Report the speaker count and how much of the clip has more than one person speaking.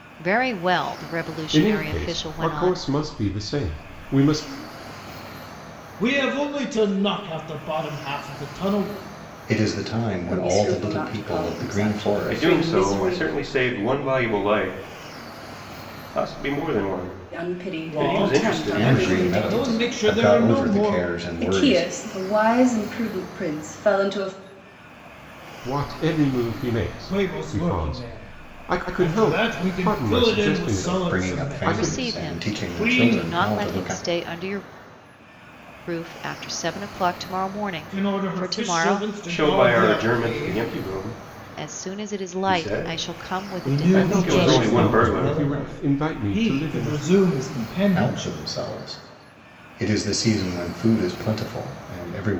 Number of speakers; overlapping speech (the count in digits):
6, about 44%